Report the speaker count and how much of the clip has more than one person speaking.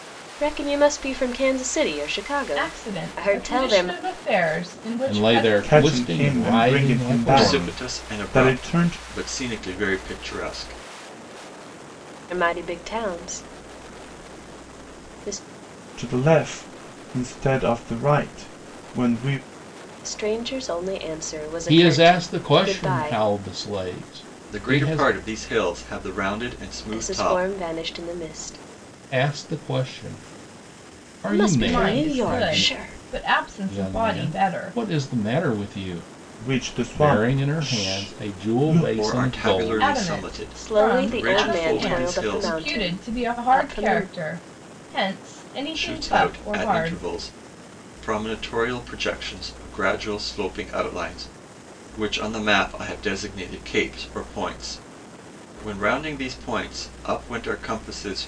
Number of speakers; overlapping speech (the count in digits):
5, about 33%